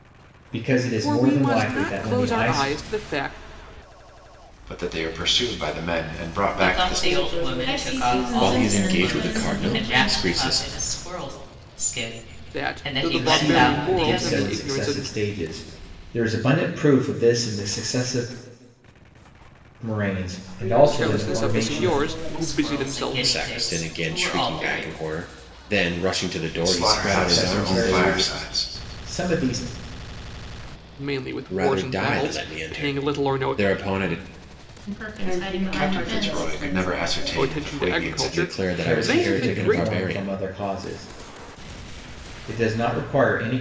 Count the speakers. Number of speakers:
7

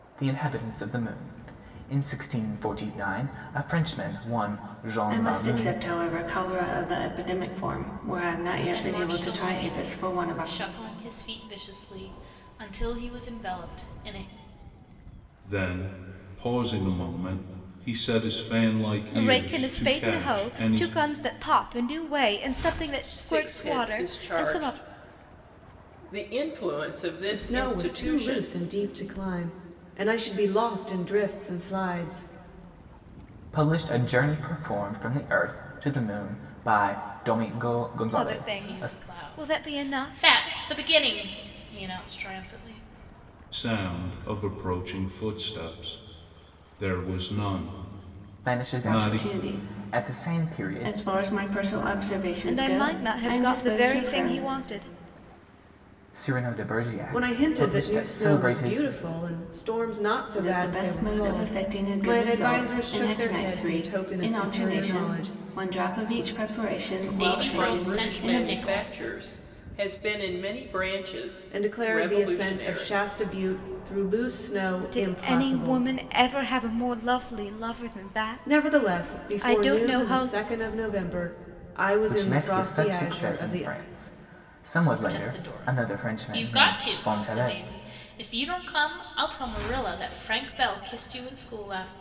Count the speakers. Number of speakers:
7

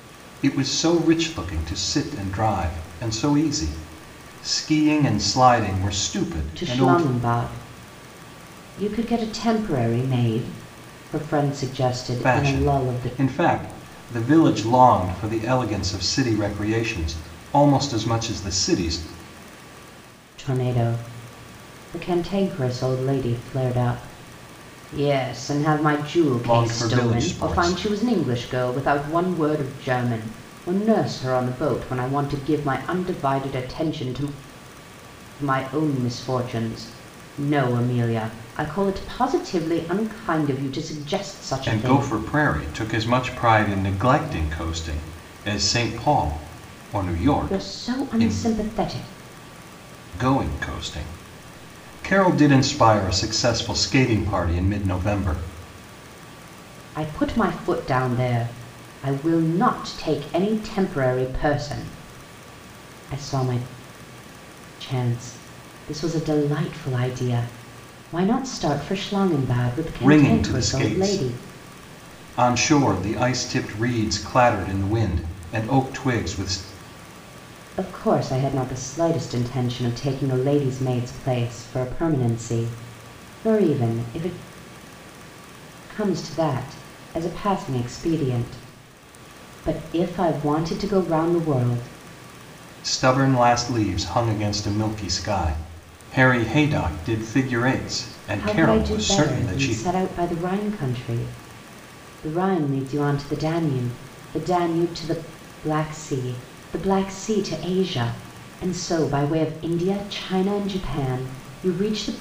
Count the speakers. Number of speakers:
2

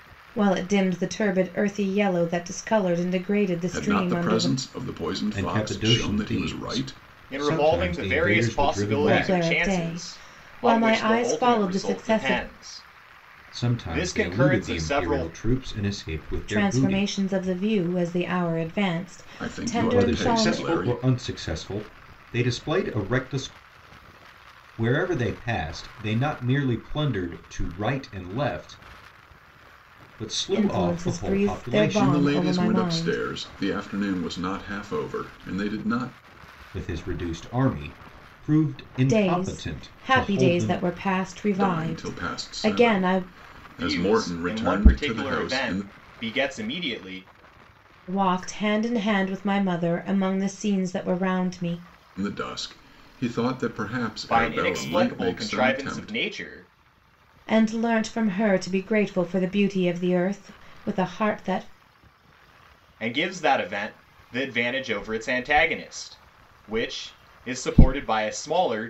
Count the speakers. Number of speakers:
4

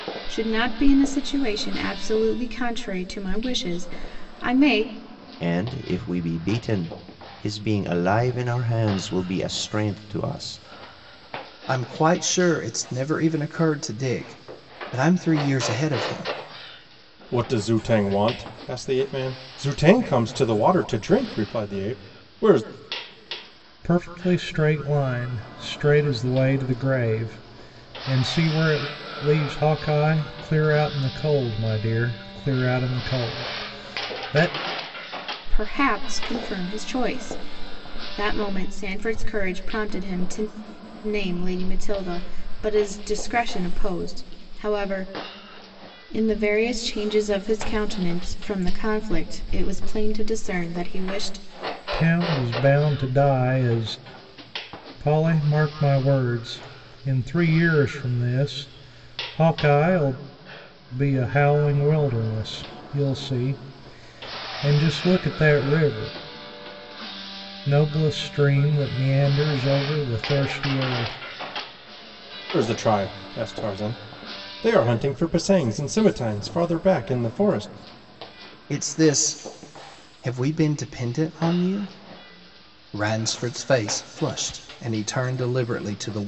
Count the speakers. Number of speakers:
5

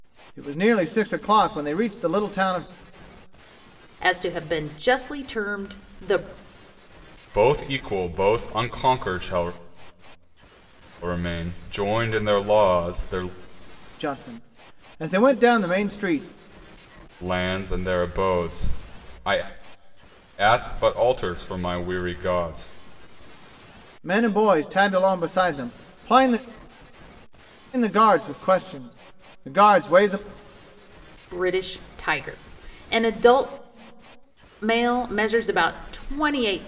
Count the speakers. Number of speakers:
3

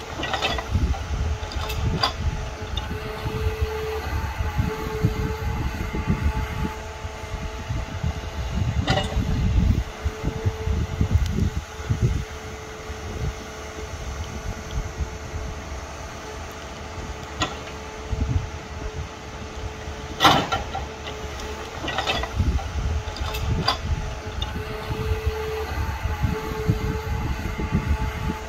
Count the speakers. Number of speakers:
0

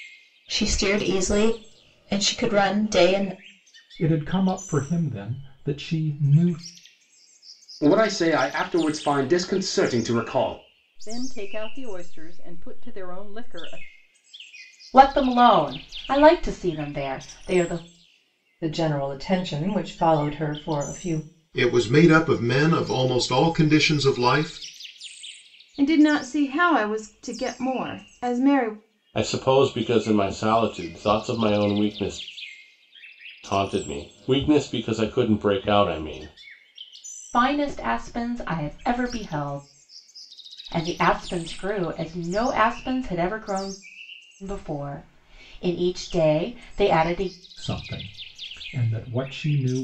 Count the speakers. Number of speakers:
9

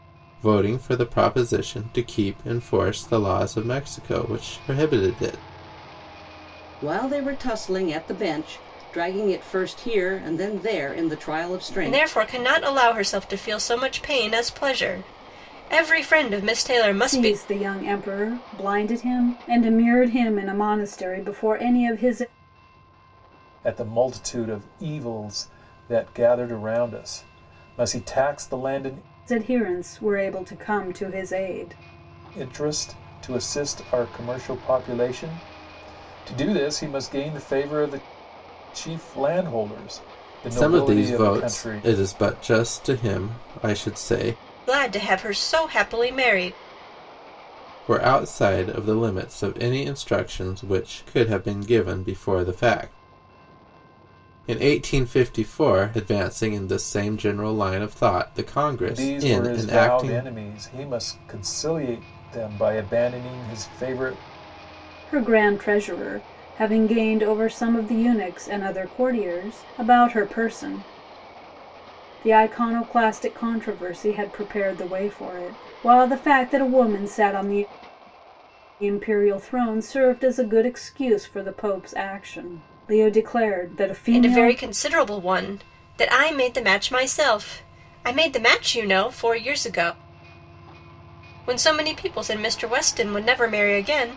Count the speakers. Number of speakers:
5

